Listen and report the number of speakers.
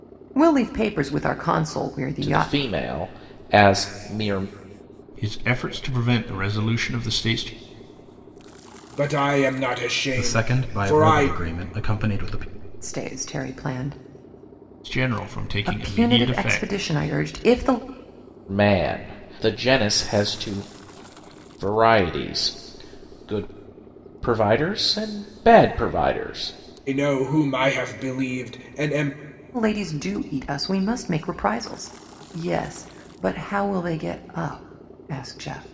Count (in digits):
5